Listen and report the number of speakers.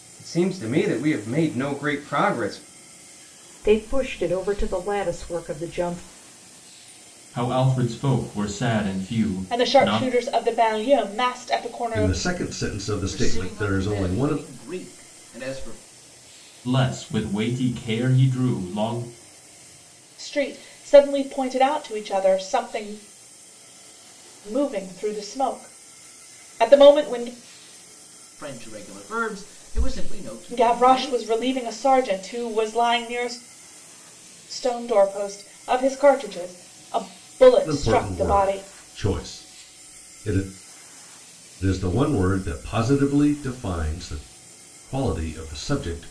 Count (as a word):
six